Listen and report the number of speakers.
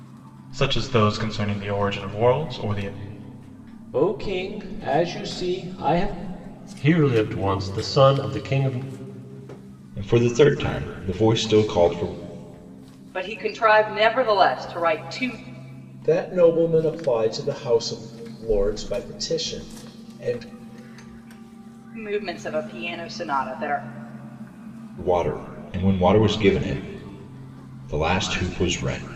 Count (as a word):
six